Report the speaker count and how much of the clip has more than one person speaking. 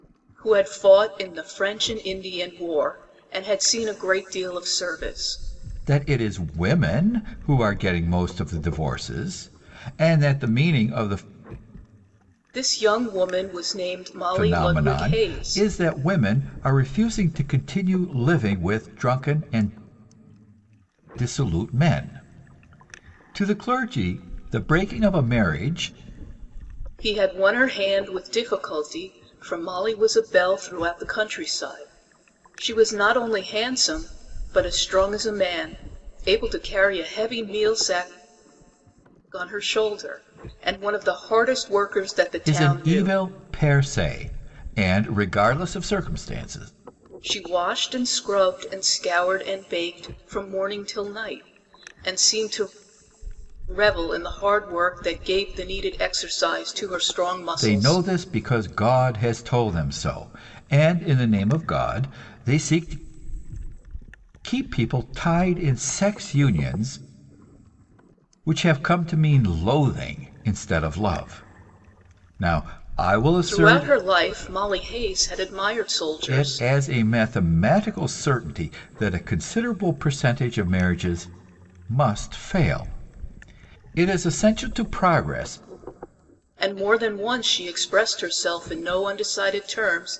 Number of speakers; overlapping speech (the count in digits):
2, about 4%